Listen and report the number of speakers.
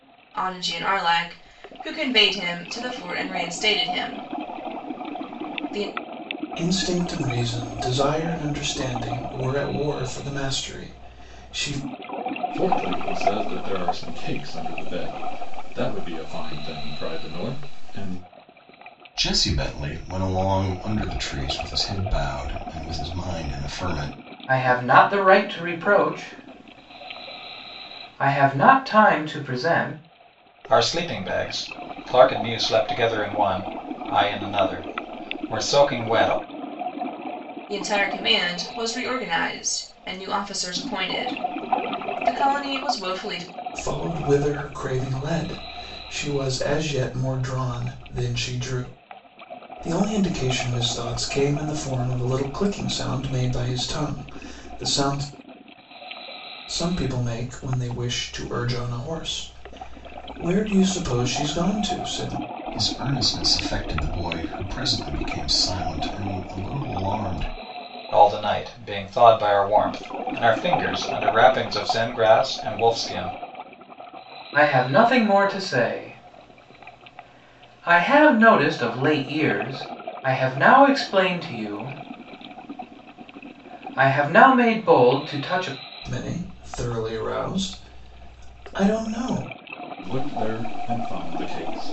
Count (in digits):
6